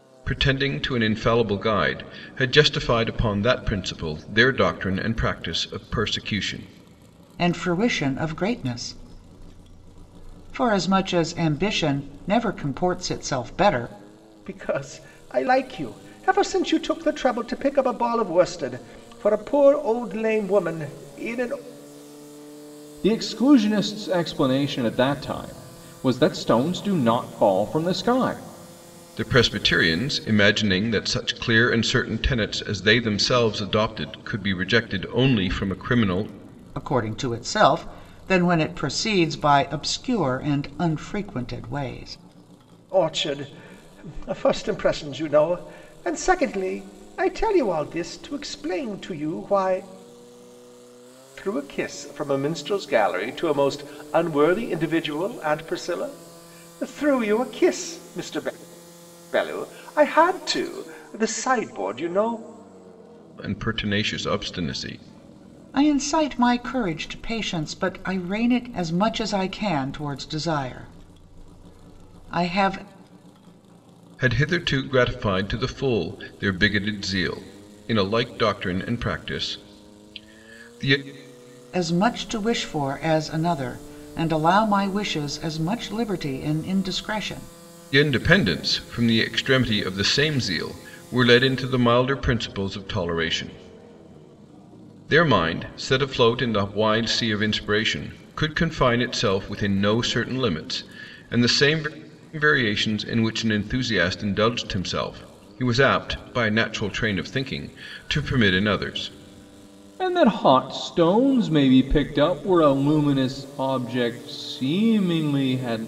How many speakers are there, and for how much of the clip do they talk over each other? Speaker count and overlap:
4, no overlap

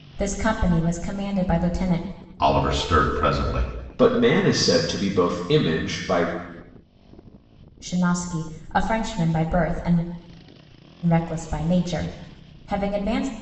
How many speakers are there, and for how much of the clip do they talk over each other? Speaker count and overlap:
3, no overlap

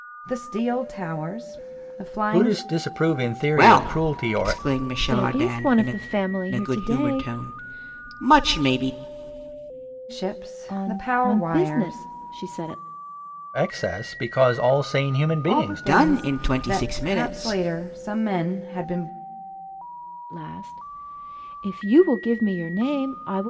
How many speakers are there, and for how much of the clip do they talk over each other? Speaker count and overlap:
4, about 28%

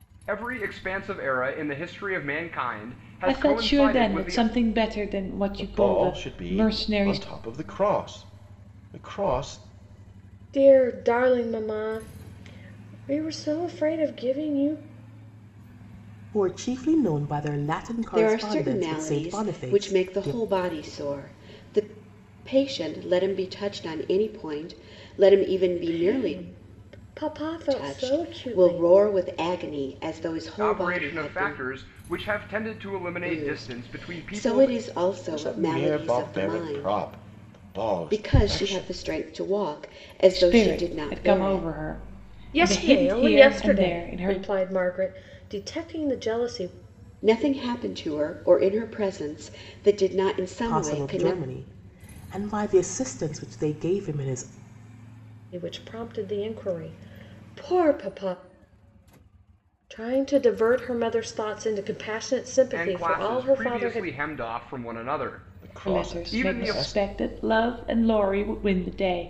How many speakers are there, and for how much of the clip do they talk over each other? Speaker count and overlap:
6, about 28%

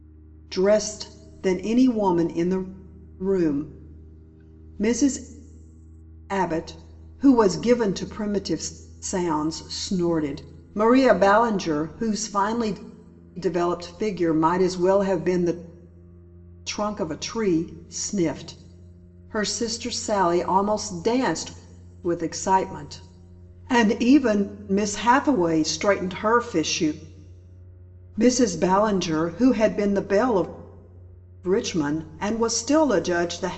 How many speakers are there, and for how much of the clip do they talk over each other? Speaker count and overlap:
1, no overlap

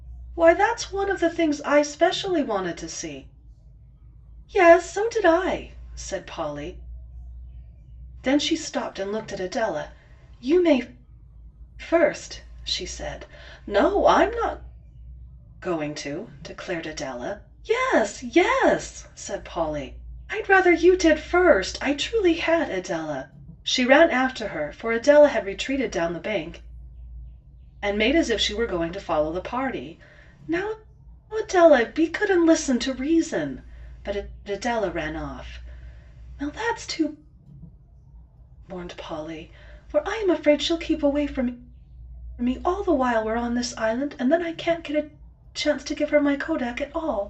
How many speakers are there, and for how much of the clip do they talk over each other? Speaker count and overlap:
1, no overlap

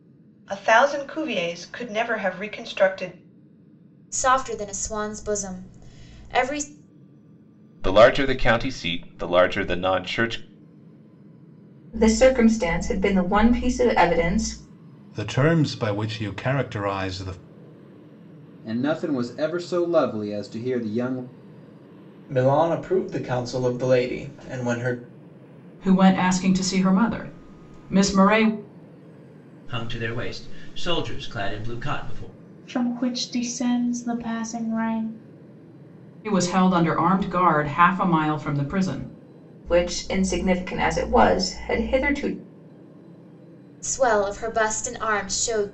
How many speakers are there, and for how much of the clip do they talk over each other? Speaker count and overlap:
10, no overlap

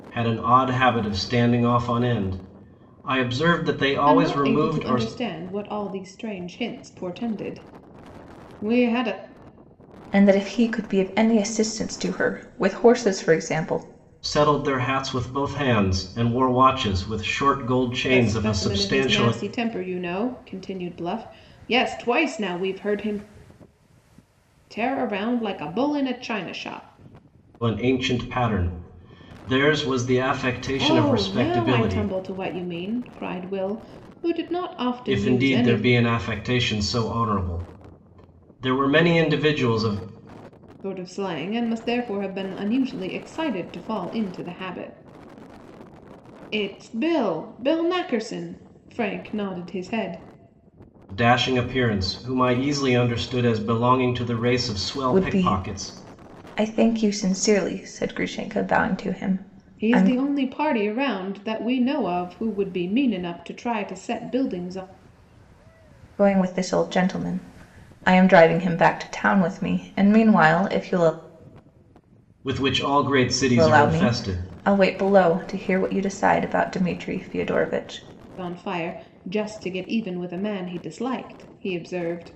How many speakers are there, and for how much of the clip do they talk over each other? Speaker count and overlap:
3, about 8%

